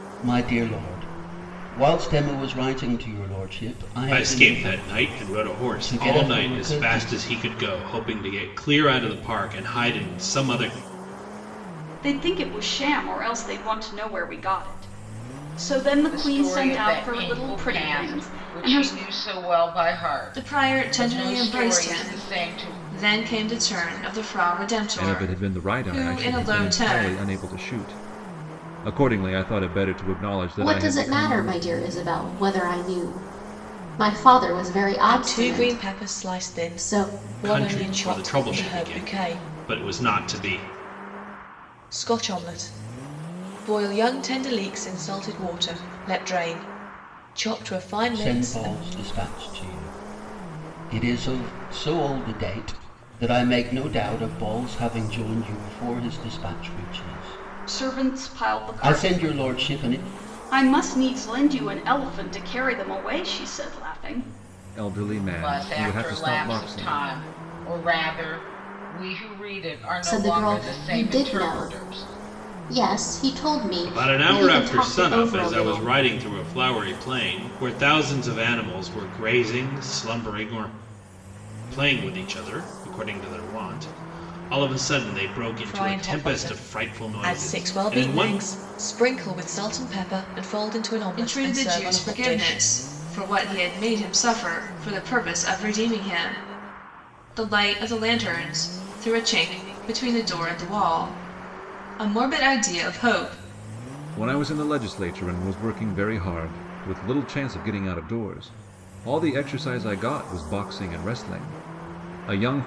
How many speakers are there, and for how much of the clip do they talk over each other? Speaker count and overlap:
eight, about 26%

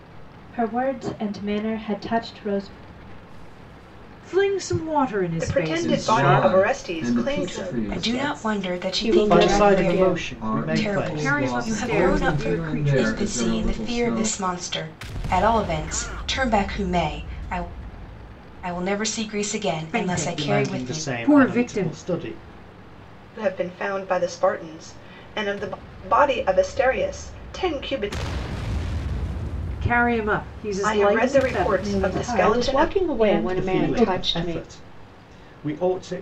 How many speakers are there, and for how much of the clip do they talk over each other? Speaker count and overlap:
eight, about 41%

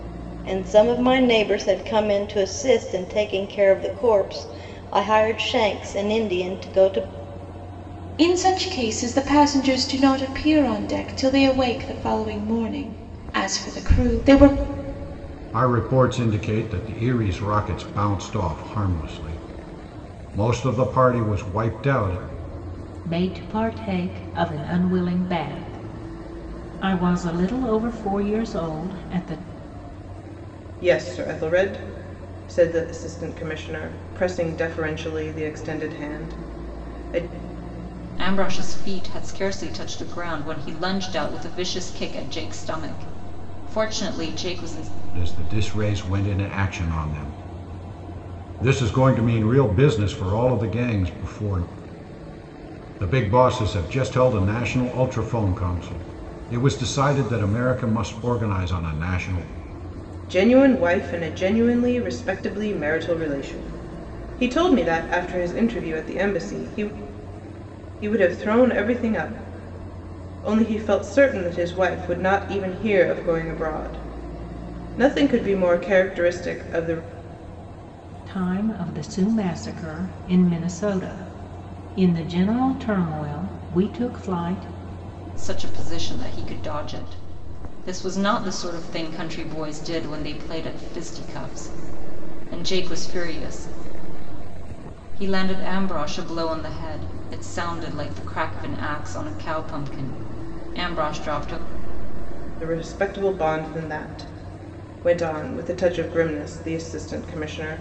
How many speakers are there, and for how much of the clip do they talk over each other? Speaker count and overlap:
six, no overlap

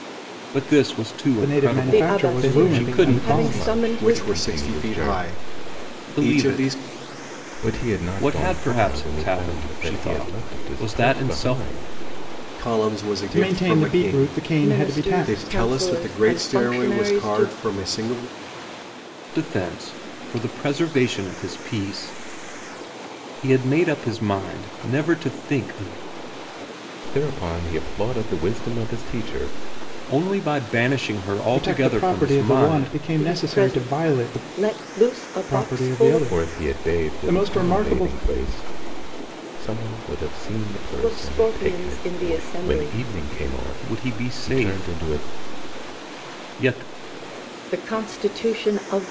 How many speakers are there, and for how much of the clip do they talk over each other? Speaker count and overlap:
five, about 45%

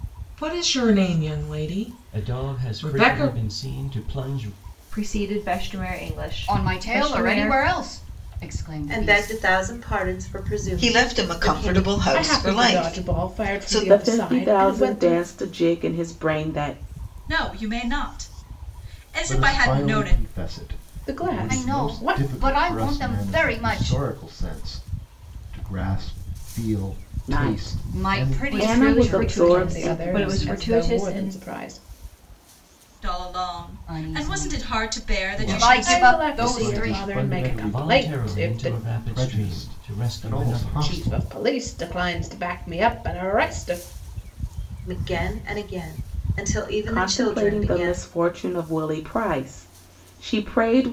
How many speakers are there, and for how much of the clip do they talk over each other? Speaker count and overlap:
ten, about 47%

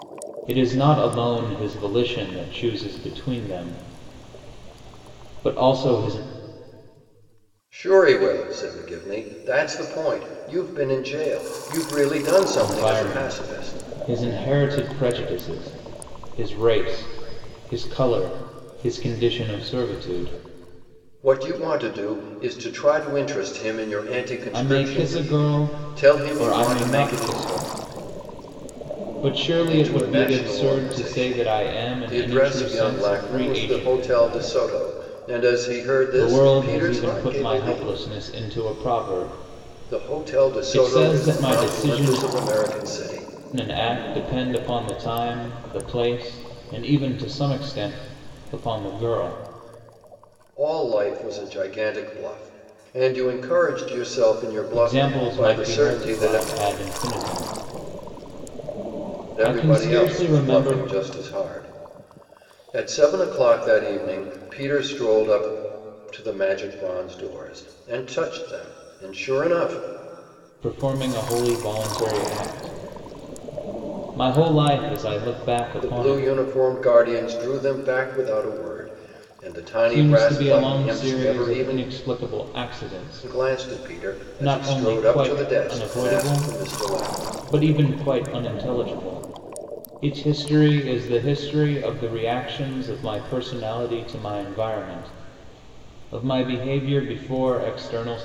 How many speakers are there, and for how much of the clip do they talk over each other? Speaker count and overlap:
two, about 23%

